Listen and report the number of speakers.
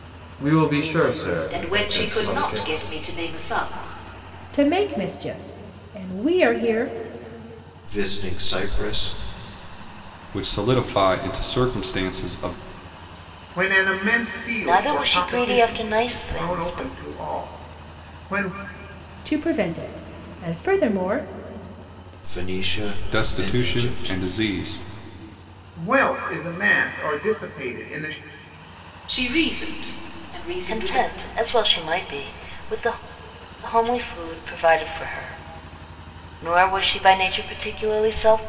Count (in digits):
7